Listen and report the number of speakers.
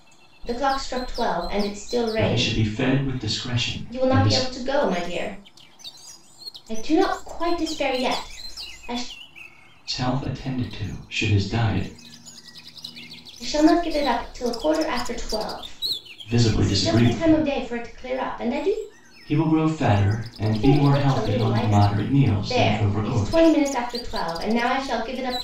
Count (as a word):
two